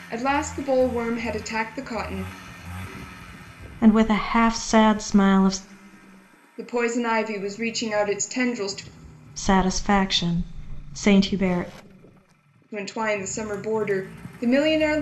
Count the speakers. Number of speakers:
2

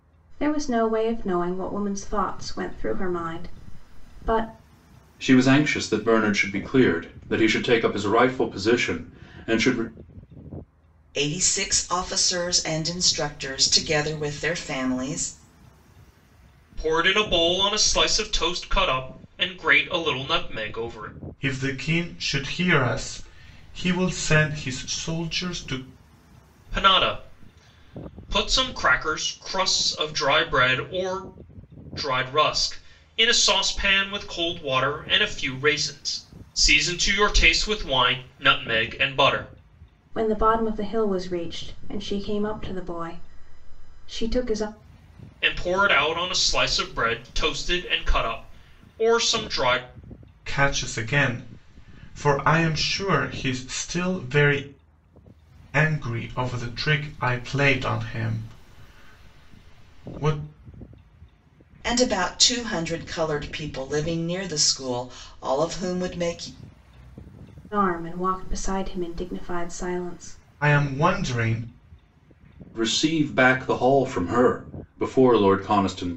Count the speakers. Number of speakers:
5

